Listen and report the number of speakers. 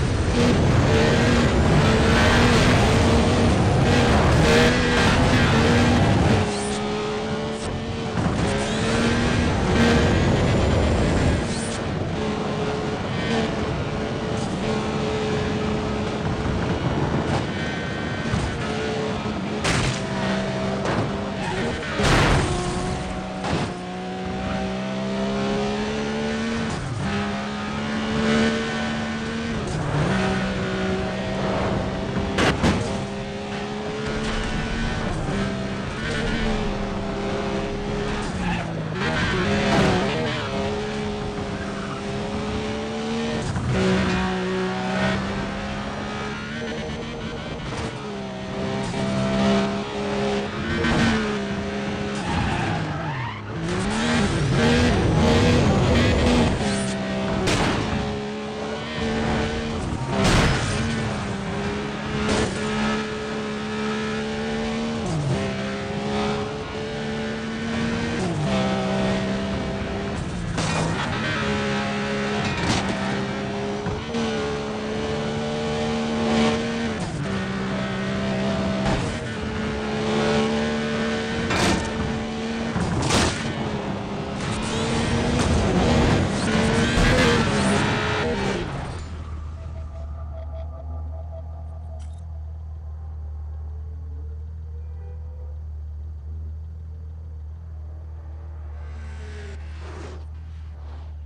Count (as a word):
zero